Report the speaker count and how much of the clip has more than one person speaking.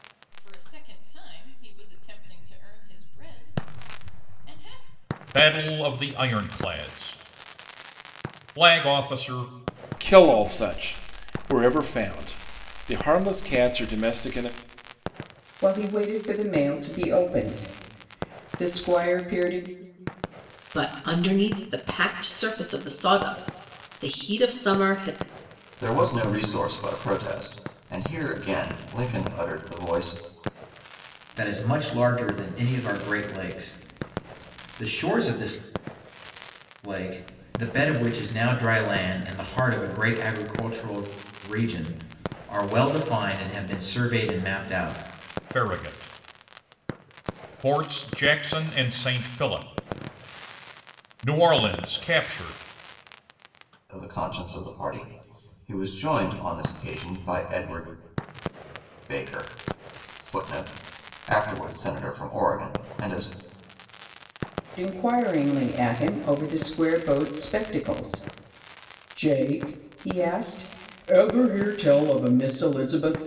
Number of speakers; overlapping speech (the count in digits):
7, no overlap